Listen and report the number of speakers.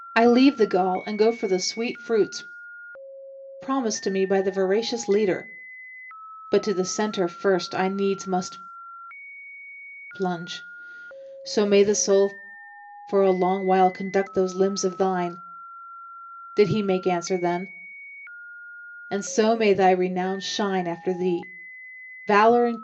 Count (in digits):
1